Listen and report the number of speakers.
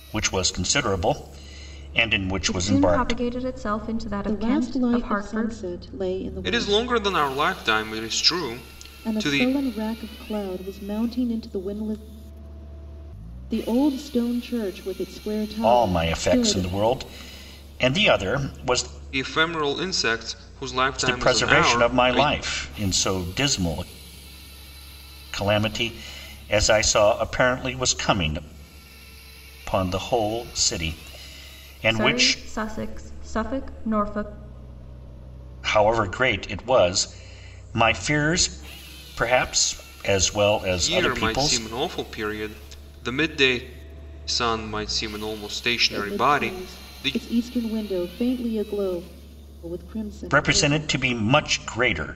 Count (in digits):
4